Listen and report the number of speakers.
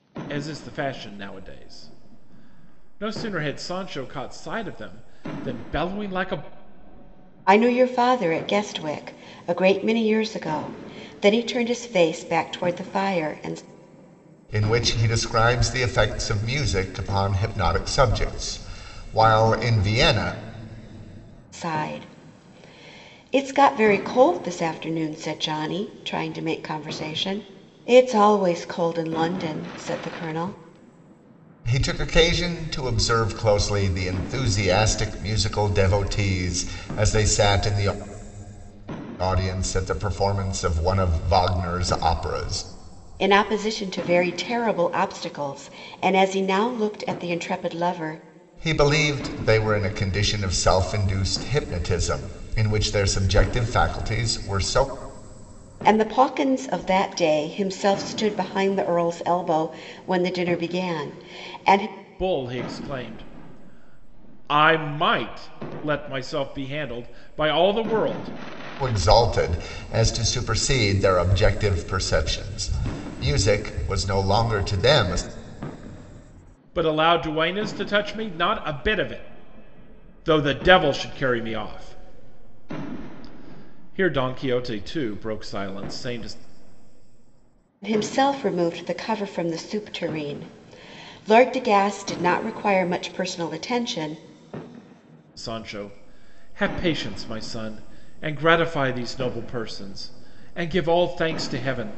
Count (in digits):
3